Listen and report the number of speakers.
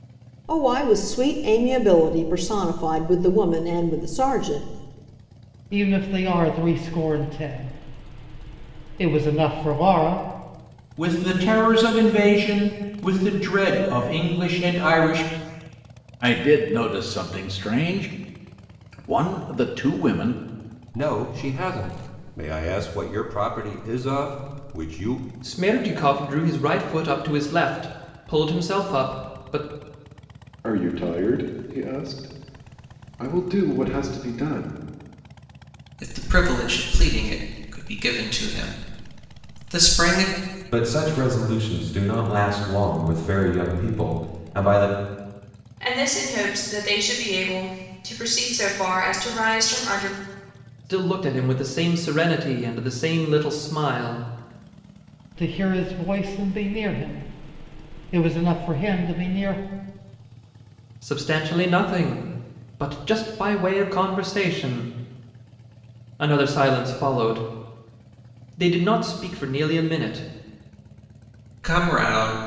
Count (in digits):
10